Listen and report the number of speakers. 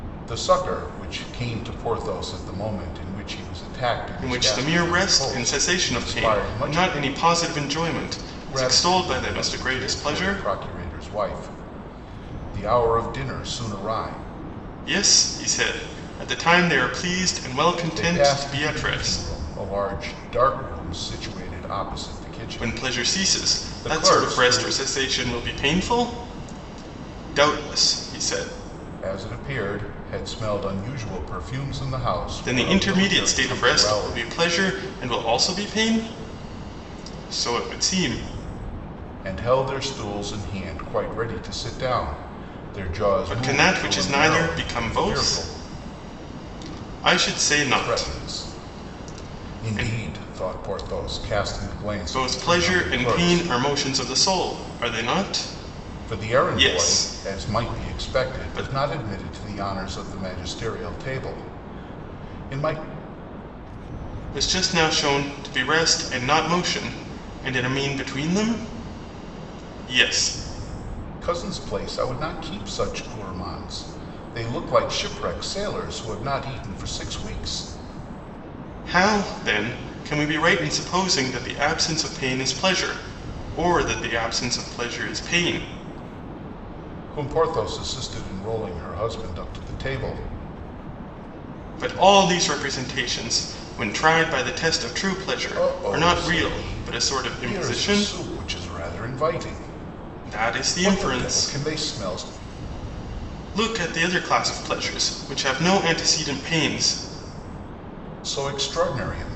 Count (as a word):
two